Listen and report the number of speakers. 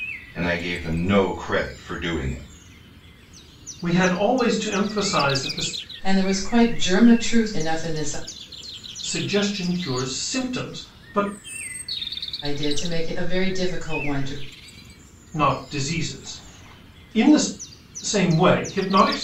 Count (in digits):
3